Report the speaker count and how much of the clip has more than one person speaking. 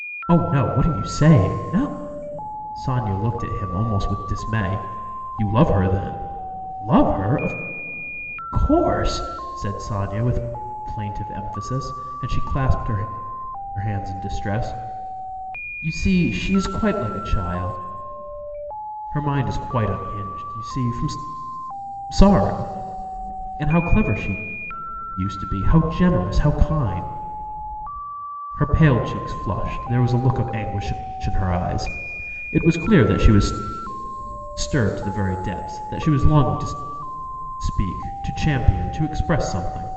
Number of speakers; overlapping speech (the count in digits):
1, no overlap